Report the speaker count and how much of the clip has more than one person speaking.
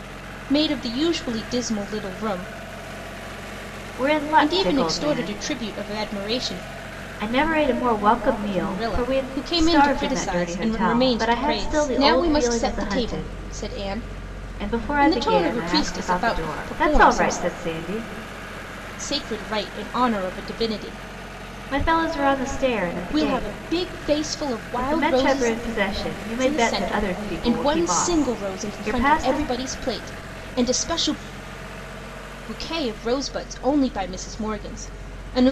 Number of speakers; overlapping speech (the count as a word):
two, about 36%